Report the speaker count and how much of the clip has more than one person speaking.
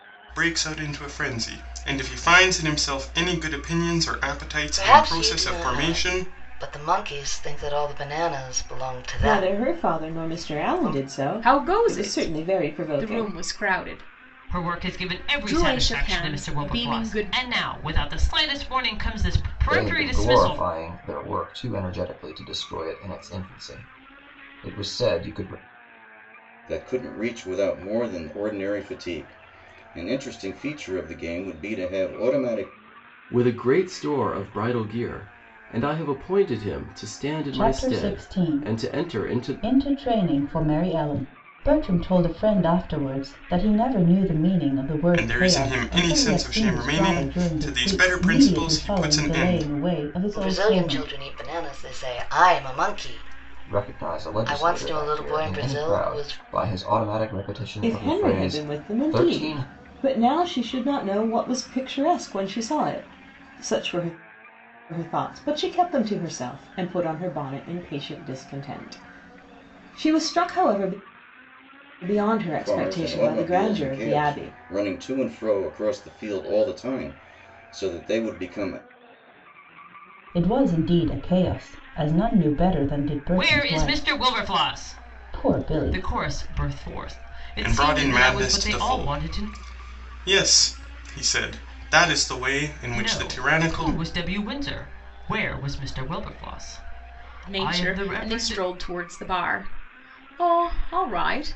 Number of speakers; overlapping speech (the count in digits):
9, about 30%